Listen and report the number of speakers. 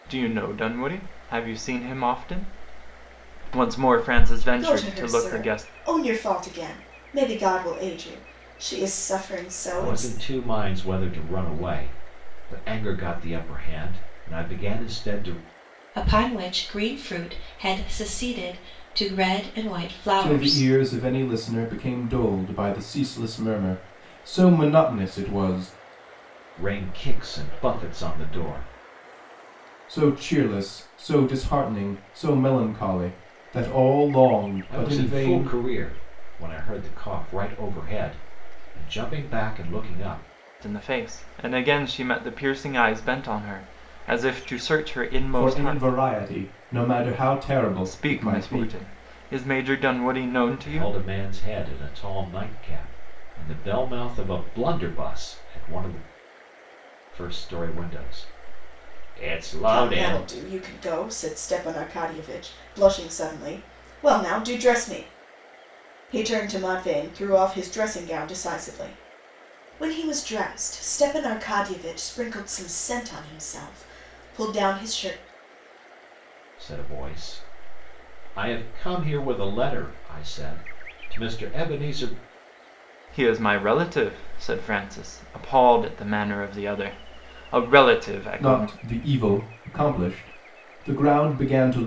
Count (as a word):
five